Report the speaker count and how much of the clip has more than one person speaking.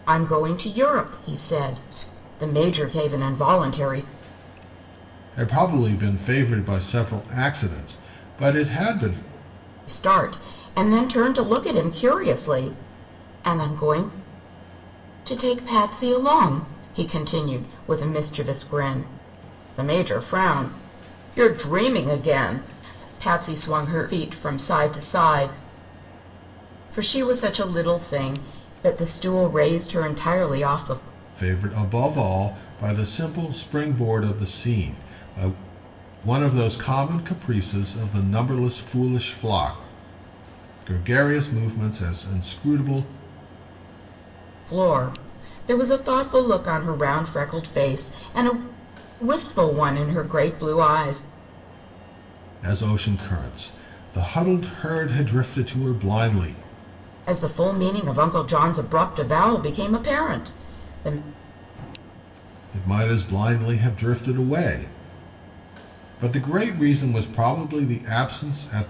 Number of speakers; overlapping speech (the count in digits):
2, no overlap